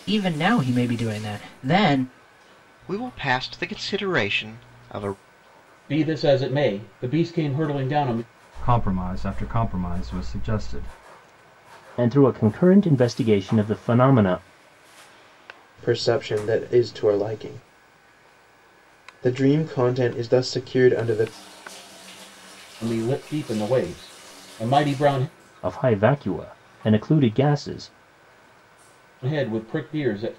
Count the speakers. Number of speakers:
six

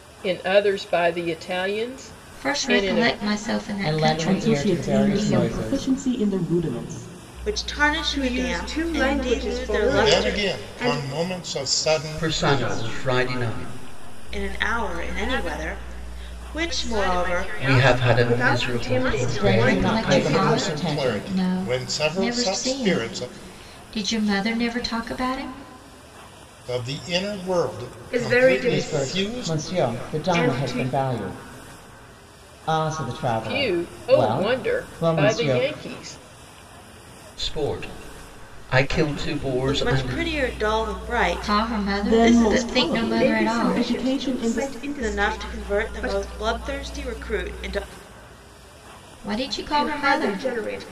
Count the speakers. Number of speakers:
nine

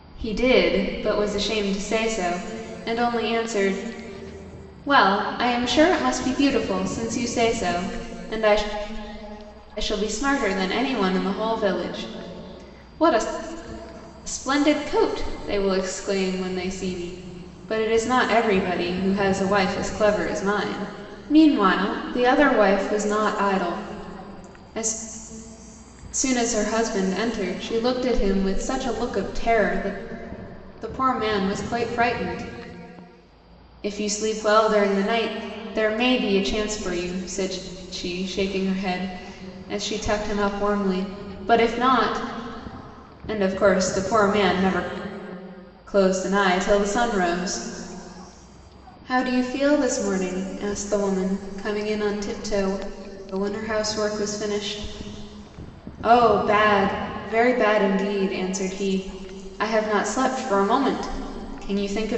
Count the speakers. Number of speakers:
one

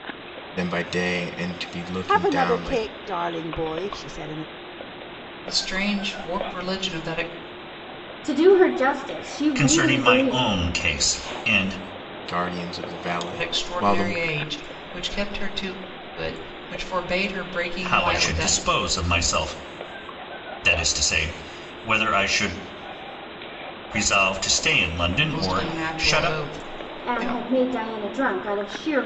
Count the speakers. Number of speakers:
five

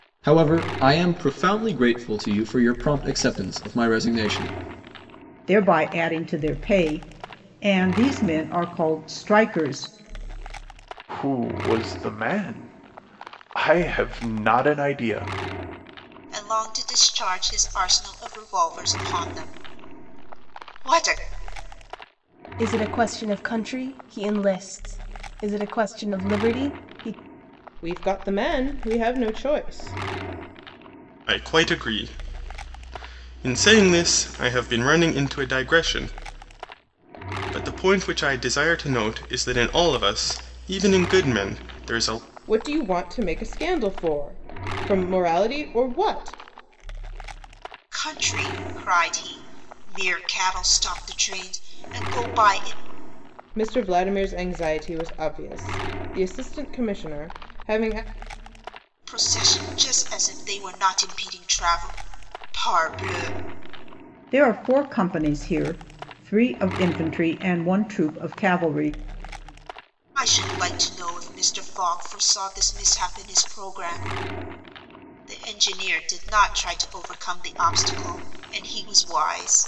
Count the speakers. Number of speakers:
seven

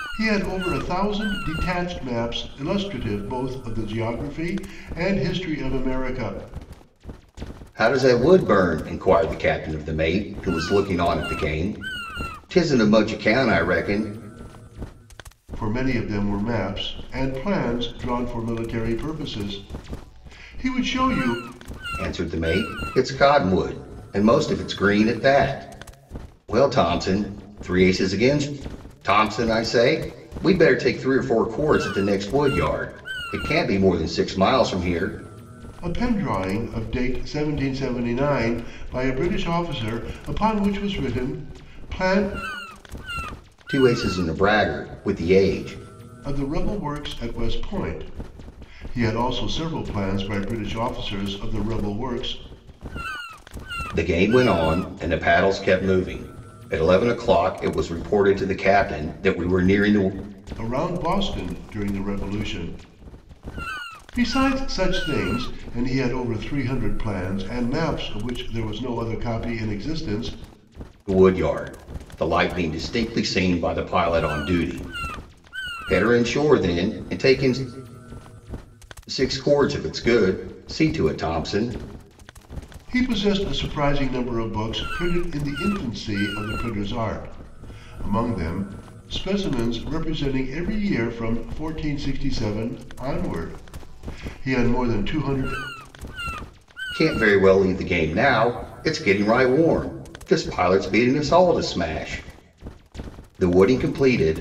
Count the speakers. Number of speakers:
two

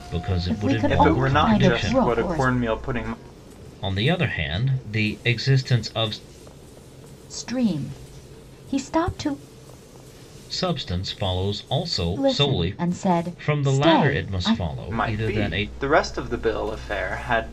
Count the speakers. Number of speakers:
three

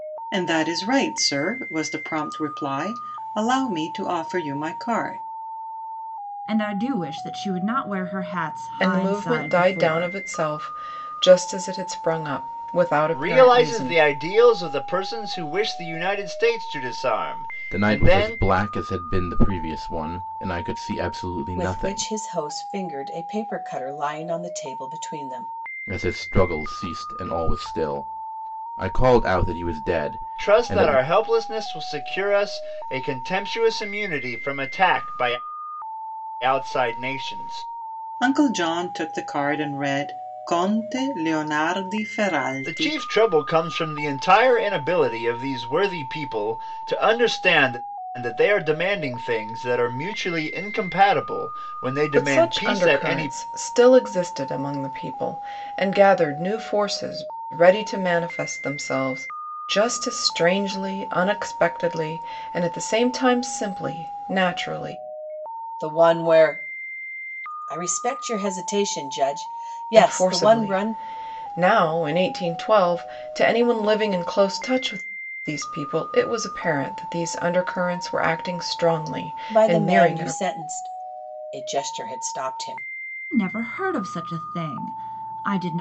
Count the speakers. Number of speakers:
six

